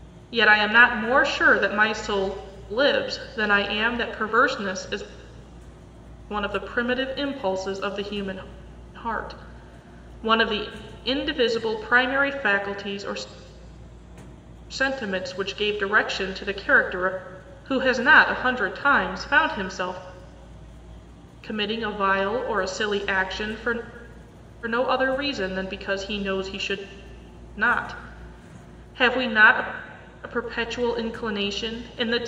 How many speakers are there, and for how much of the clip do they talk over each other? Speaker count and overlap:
1, no overlap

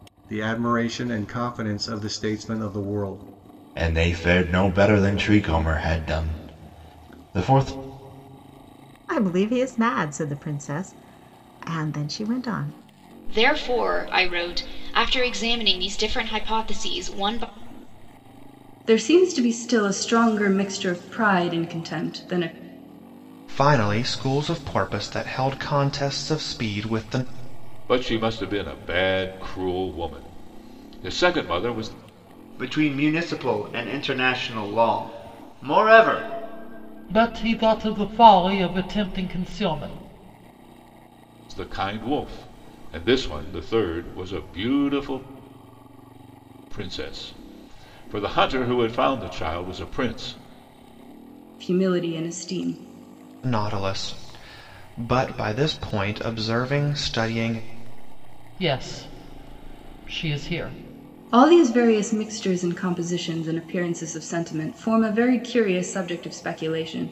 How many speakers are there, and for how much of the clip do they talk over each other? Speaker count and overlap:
9, no overlap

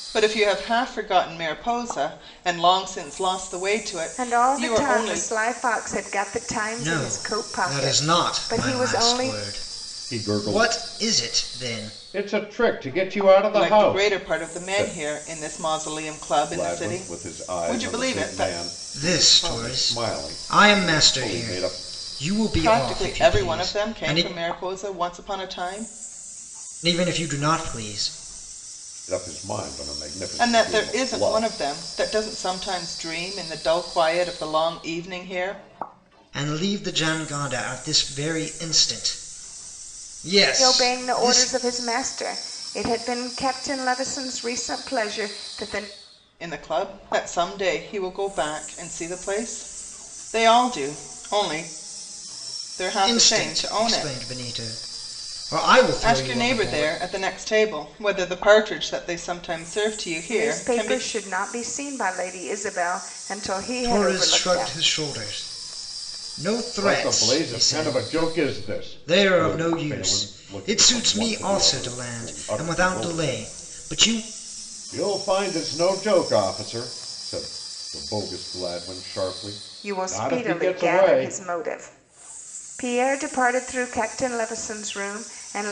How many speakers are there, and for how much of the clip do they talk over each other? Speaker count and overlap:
4, about 32%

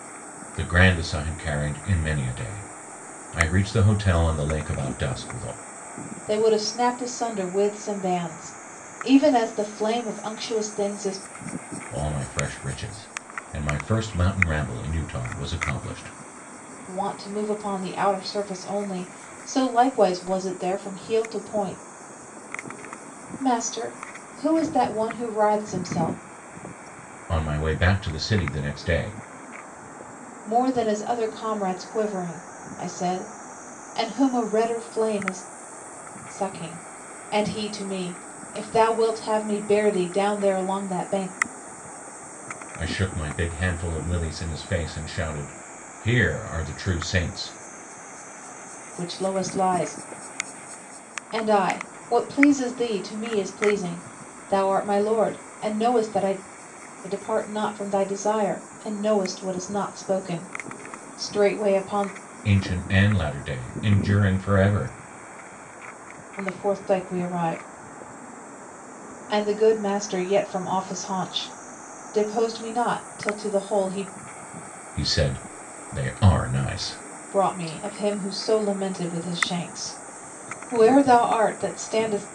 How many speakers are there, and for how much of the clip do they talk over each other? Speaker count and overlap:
2, no overlap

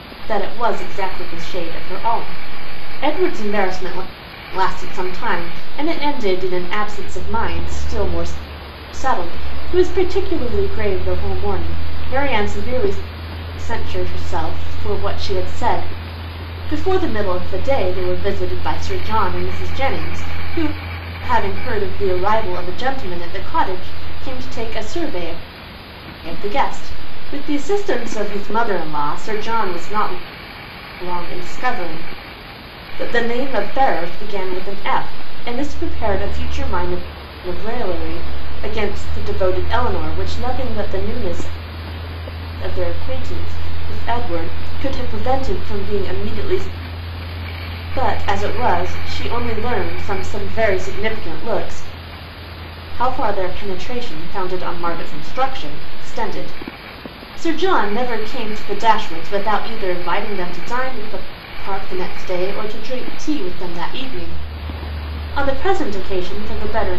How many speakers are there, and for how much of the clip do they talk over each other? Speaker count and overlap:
1, no overlap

